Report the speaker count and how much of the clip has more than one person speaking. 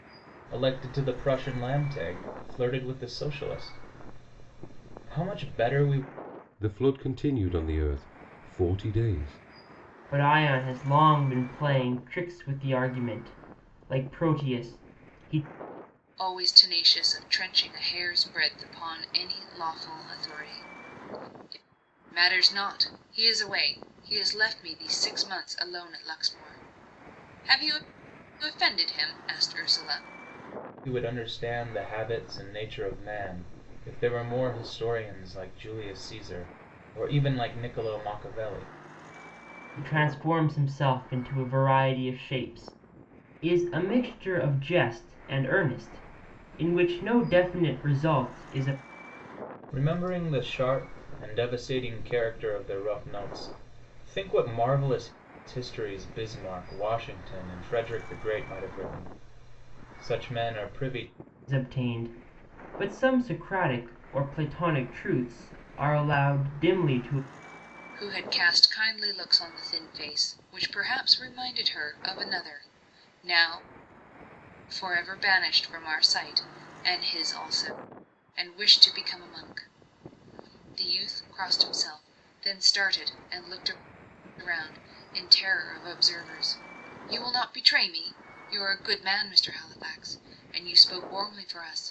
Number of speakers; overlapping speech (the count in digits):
4, no overlap